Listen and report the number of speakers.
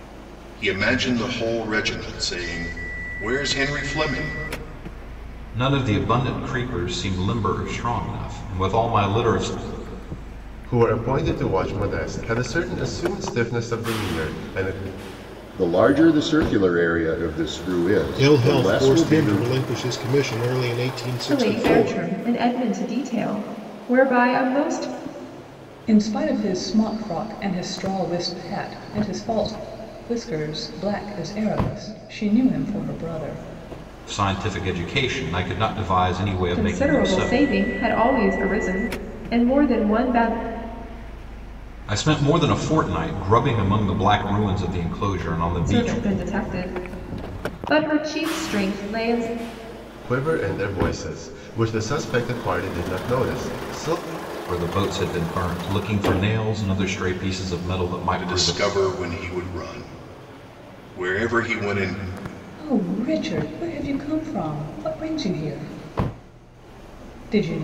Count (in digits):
7